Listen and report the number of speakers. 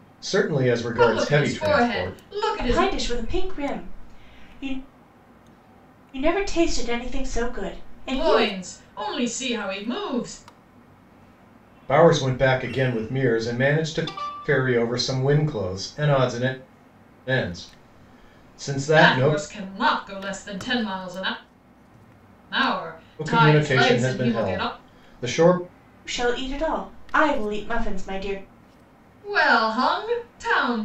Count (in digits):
3